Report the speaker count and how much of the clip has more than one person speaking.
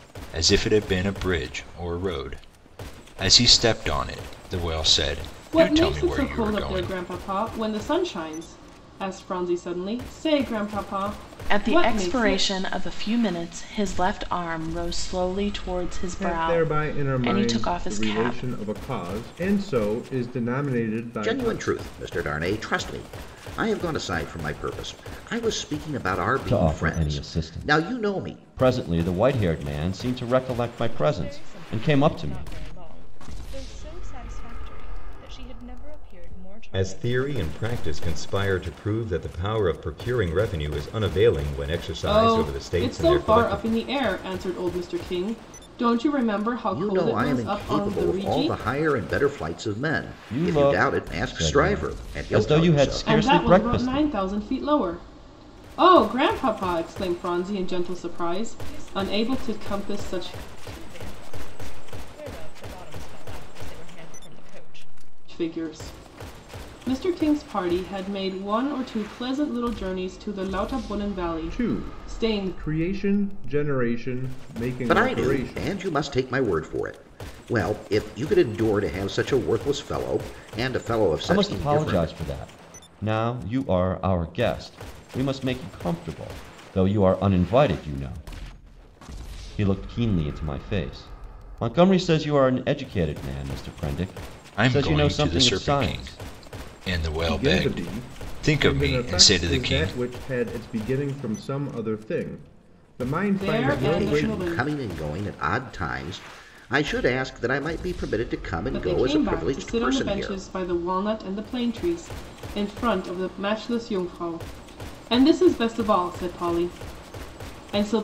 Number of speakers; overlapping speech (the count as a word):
eight, about 26%